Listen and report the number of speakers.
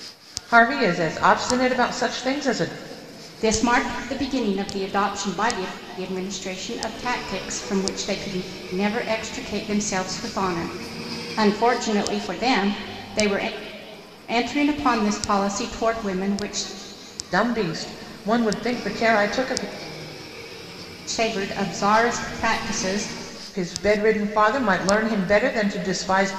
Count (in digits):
2